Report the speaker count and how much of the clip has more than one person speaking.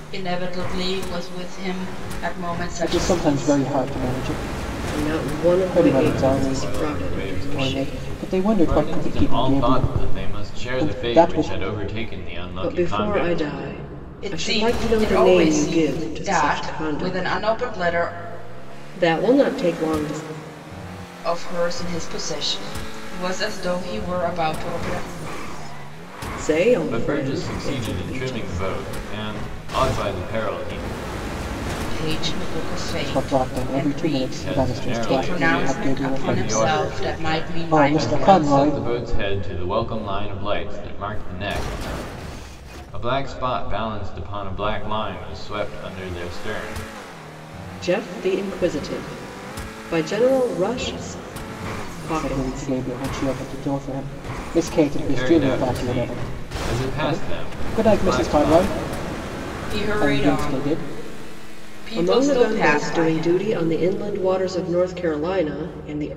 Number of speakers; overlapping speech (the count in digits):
4, about 40%